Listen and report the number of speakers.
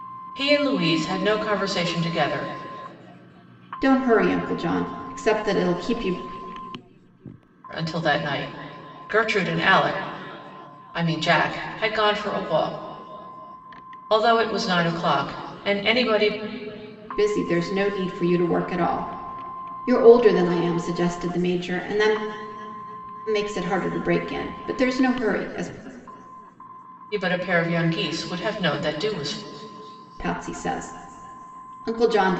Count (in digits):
2